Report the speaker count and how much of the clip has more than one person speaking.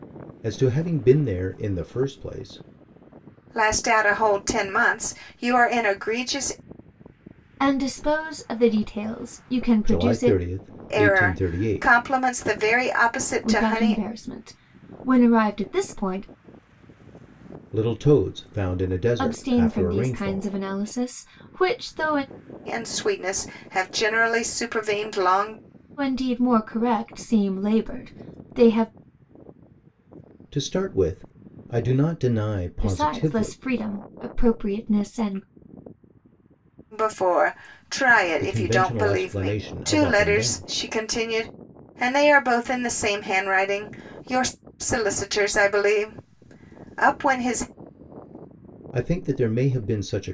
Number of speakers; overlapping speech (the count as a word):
three, about 13%